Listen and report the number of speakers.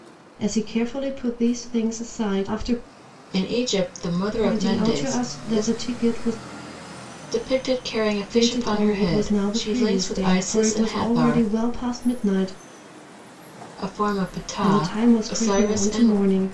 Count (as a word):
two